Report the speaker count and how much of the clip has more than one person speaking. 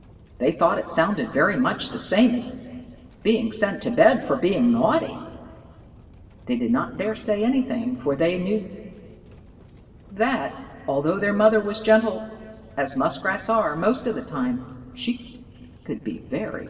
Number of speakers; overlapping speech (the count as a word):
one, no overlap